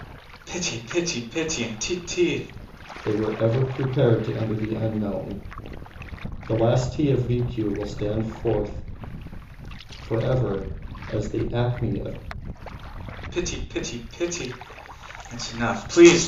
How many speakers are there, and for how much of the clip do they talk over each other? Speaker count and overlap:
two, no overlap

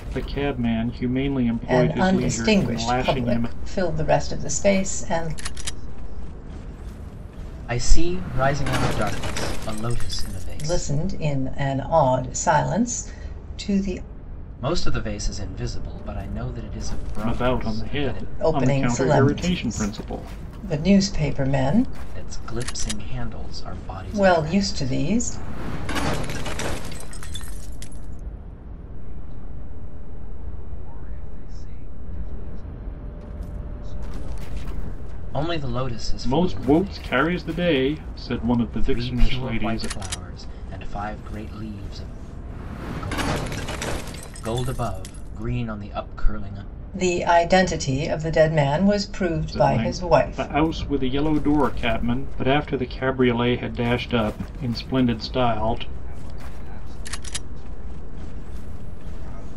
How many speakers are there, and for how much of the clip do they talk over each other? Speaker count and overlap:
four, about 34%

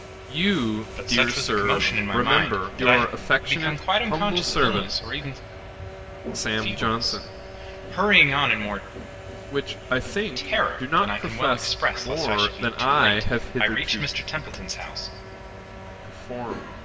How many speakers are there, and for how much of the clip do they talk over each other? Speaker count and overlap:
two, about 49%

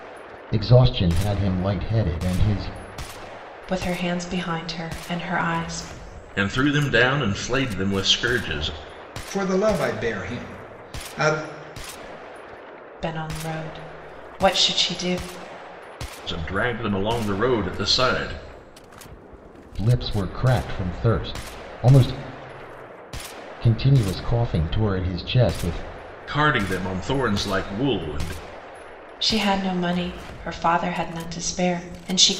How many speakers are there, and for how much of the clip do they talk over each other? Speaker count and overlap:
four, no overlap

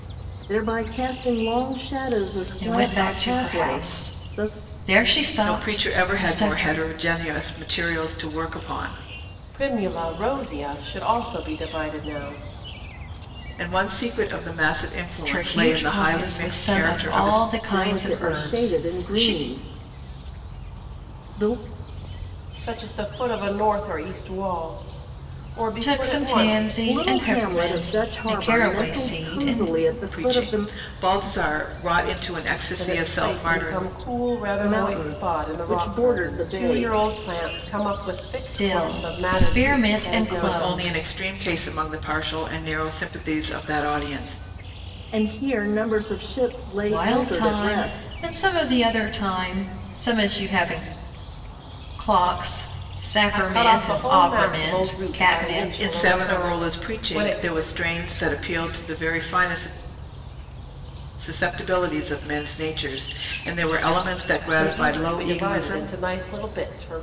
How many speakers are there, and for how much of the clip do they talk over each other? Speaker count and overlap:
four, about 37%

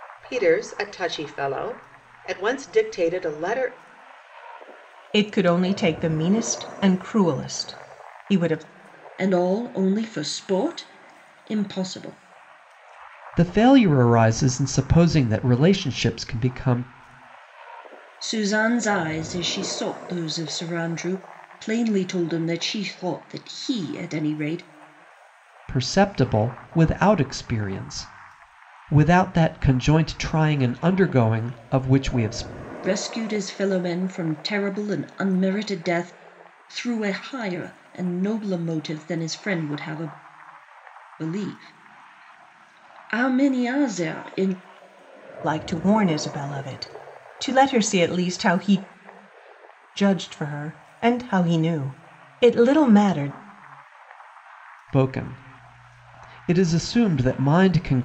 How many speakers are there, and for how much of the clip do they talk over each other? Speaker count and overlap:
four, no overlap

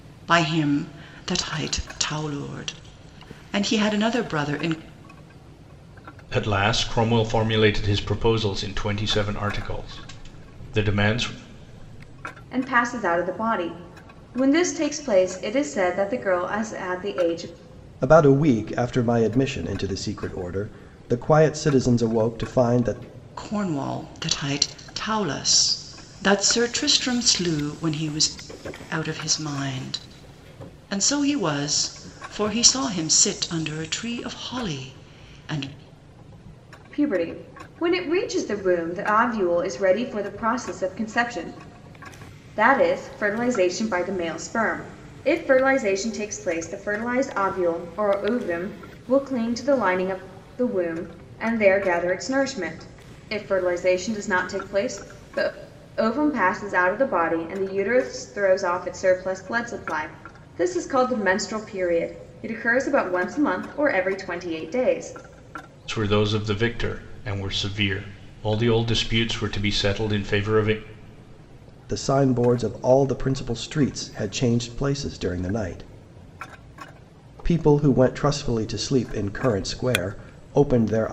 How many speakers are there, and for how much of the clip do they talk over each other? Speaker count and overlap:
four, no overlap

